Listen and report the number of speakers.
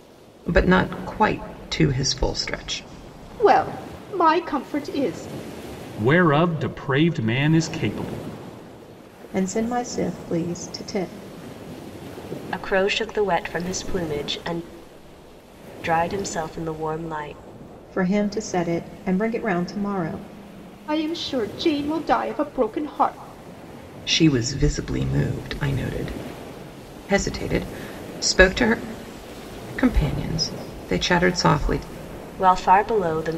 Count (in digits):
5